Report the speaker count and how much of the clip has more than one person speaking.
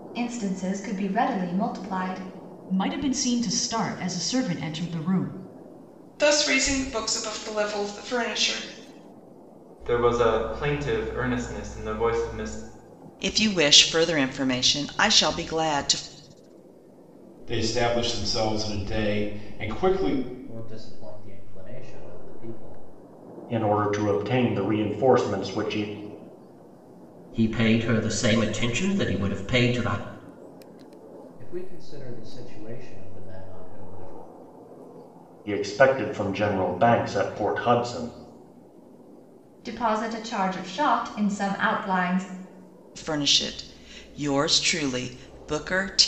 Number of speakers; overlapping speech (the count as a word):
nine, no overlap